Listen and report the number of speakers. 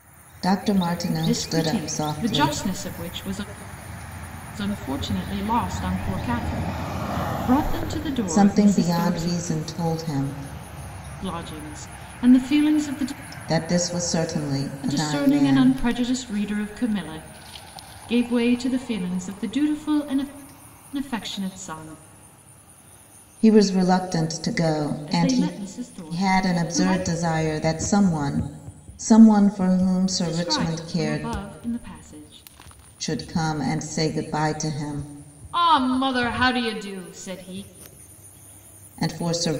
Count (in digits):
2